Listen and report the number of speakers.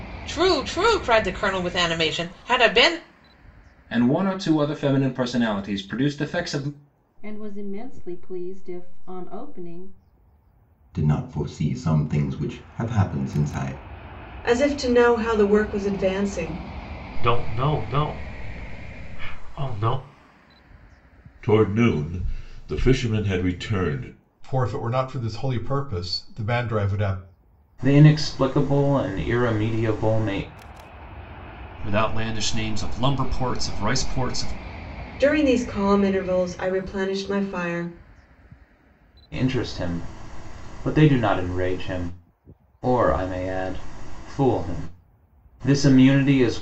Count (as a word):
ten